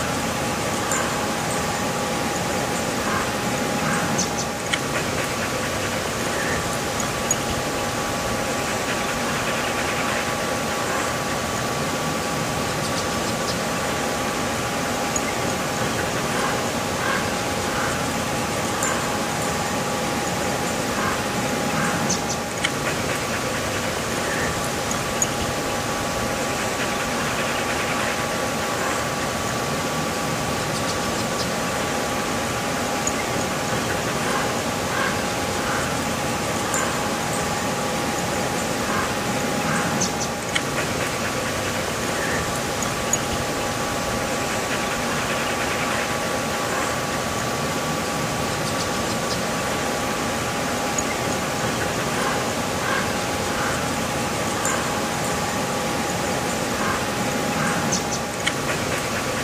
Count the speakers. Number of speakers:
zero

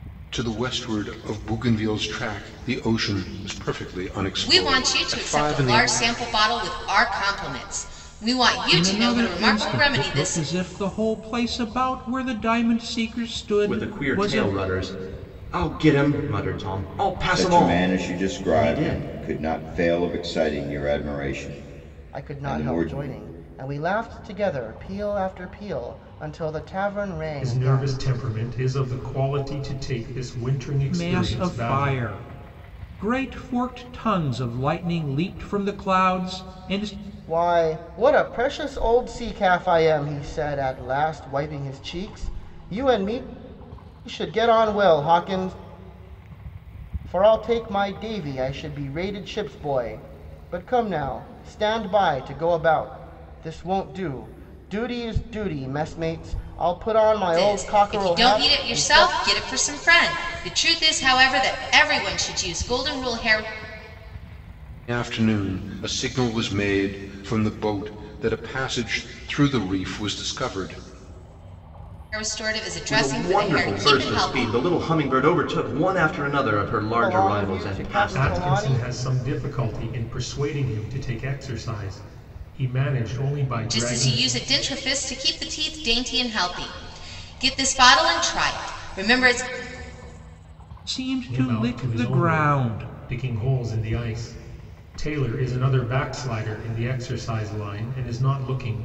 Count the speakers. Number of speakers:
seven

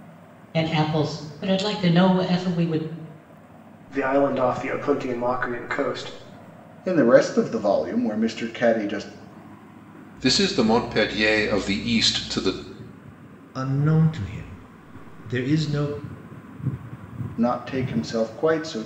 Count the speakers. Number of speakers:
five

